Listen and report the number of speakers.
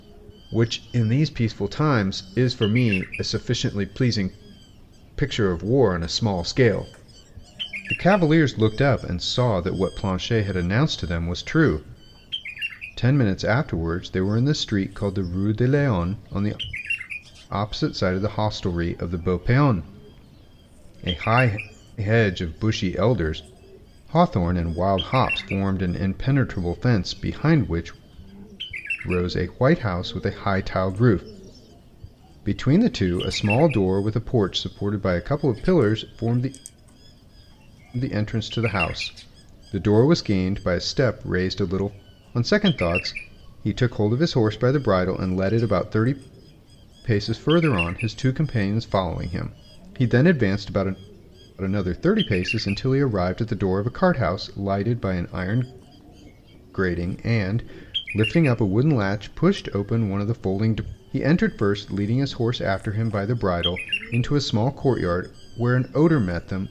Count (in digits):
1